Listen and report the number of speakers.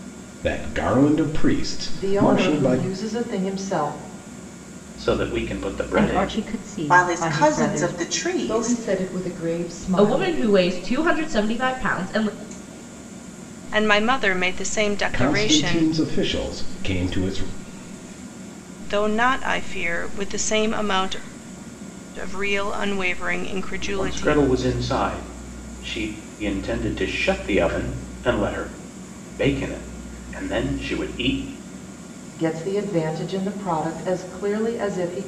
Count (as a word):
eight